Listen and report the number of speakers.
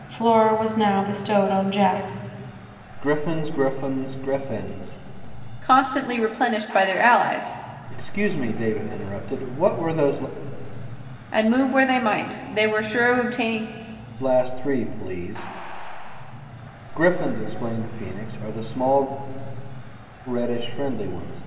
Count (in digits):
3